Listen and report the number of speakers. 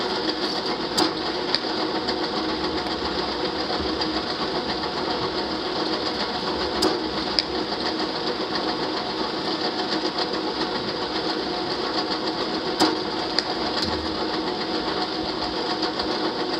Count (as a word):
zero